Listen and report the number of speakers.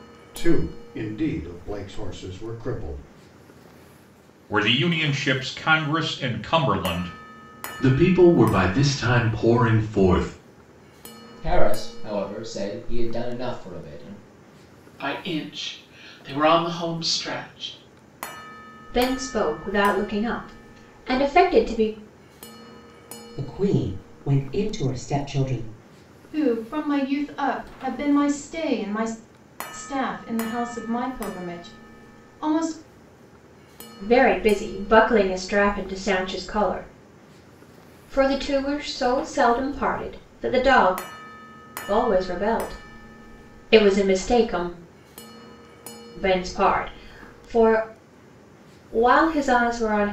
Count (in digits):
8